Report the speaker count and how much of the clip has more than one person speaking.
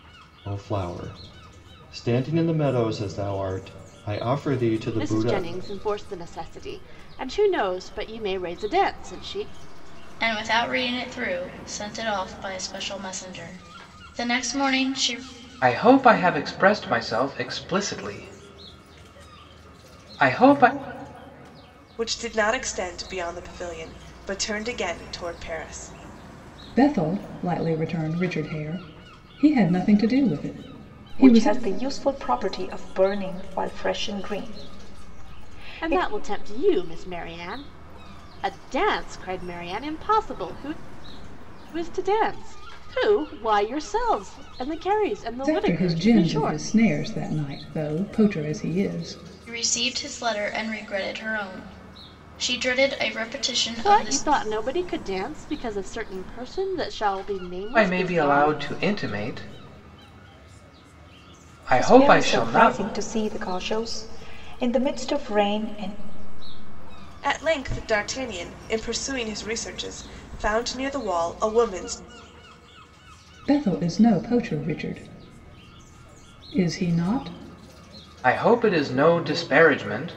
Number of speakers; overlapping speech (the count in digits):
7, about 6%